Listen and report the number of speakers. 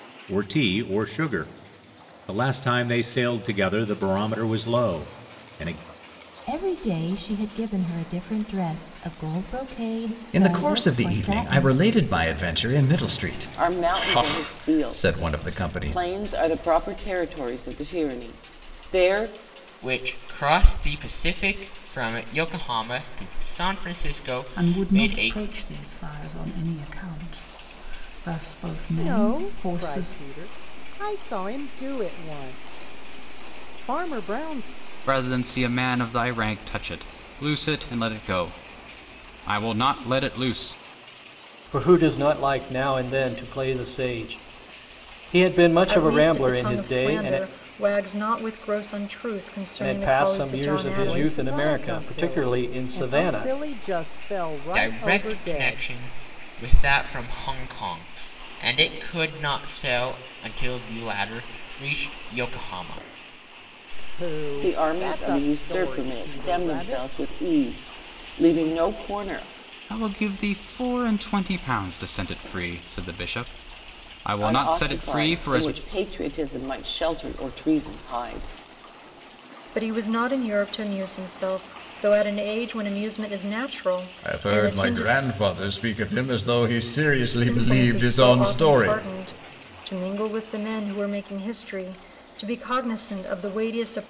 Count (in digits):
10